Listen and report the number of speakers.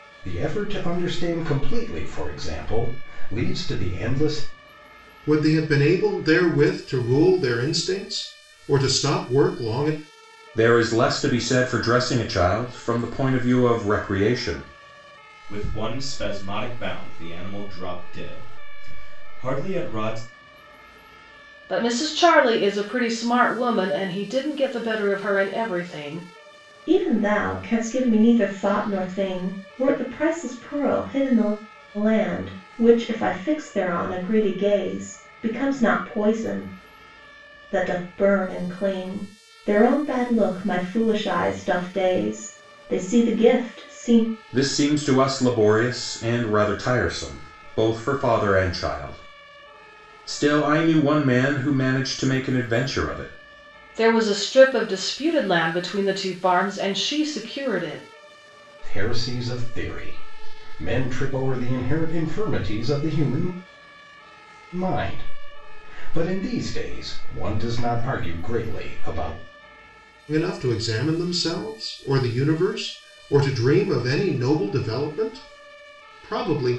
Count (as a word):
six